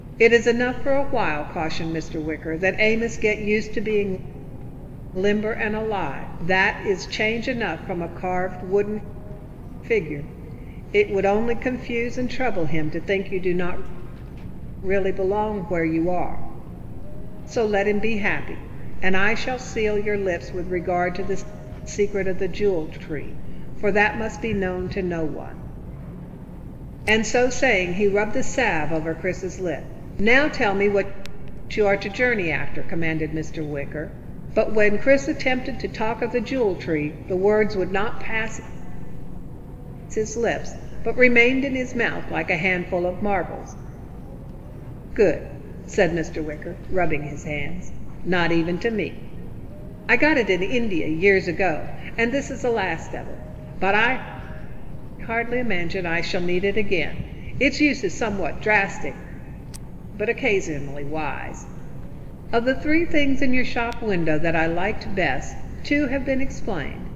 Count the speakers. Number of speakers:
1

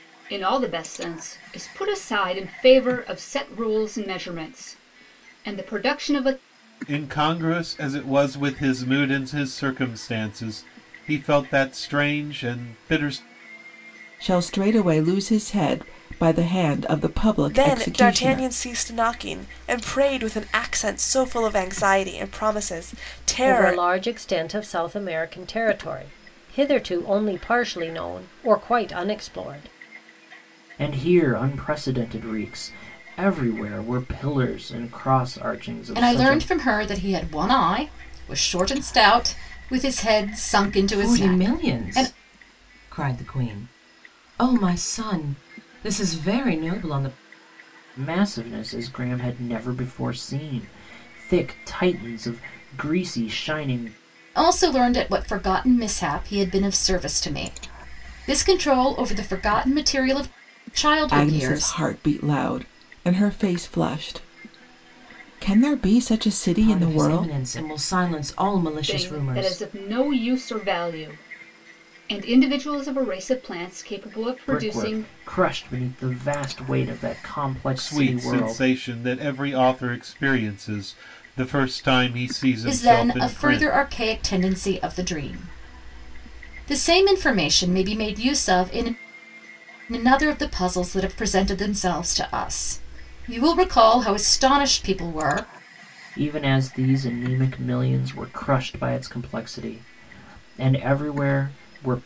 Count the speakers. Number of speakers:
8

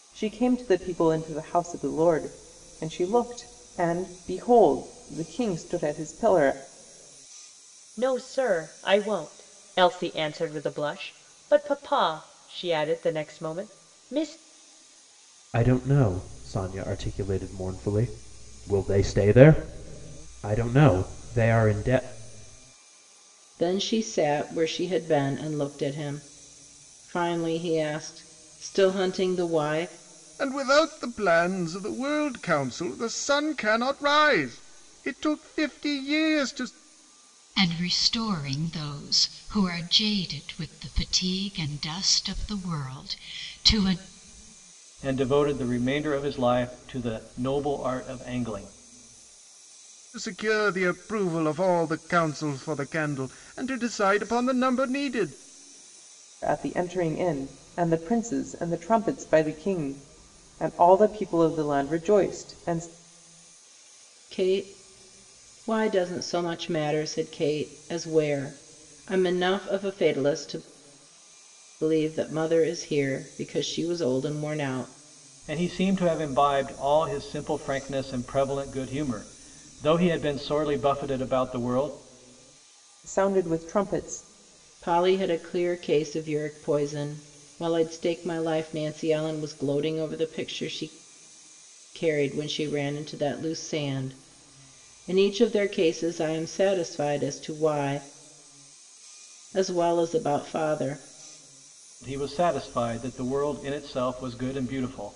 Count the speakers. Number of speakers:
7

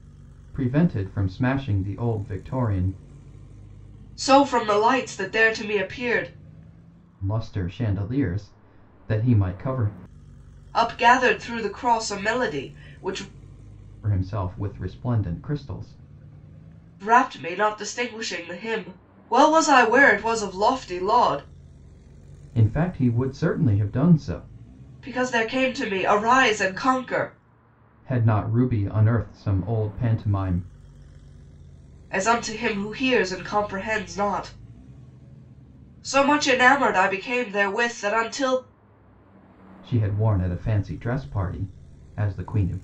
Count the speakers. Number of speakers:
2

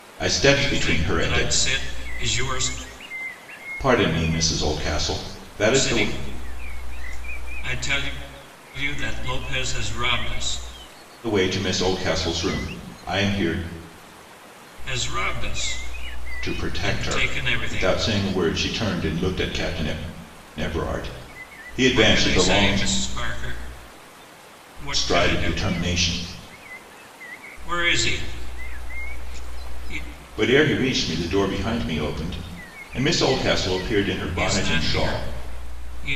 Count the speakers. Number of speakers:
2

